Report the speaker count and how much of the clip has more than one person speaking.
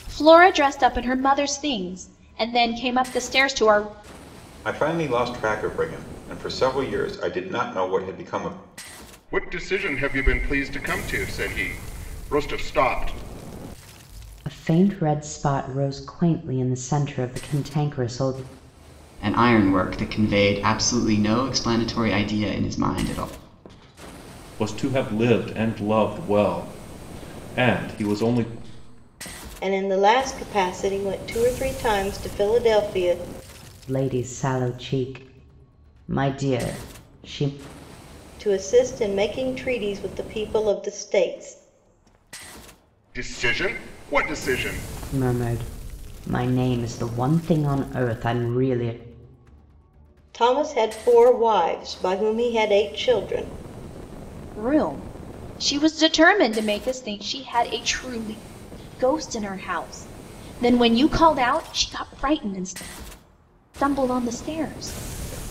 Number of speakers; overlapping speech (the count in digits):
7, no overlap